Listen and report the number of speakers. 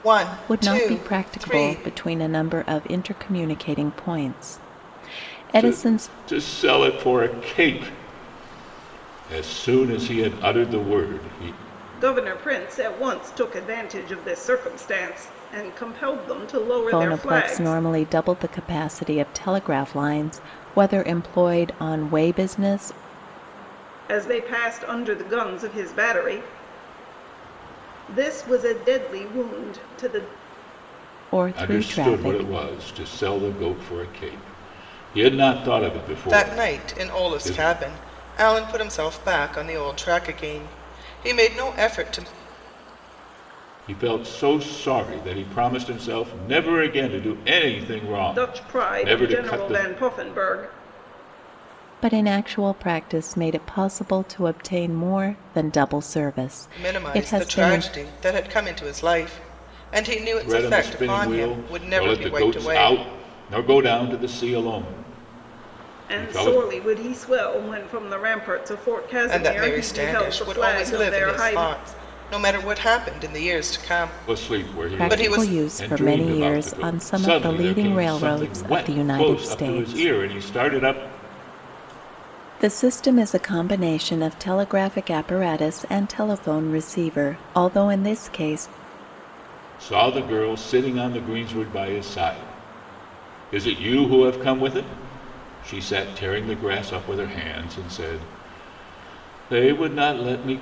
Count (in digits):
4